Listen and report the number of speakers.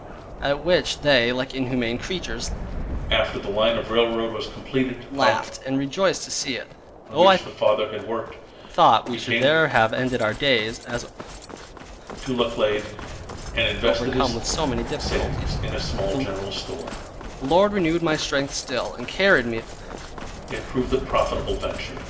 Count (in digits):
2